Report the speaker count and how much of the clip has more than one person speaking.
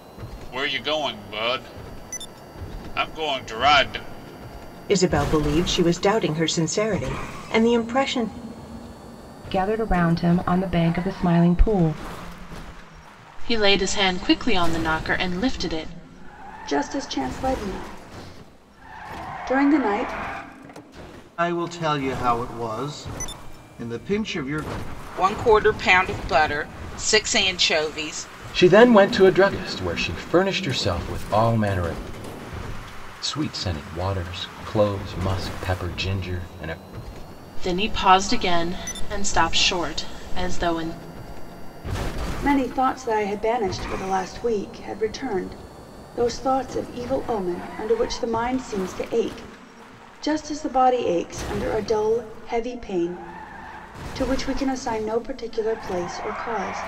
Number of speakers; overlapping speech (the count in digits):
8, no overlap